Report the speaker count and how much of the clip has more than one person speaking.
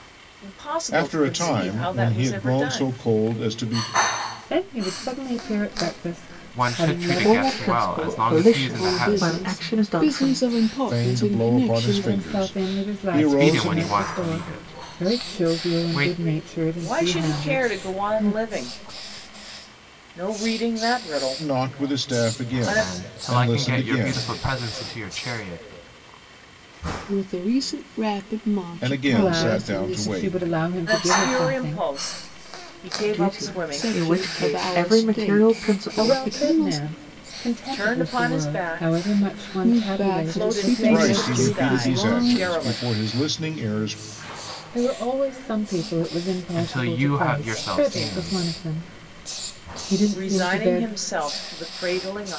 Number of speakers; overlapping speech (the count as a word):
six, about 57%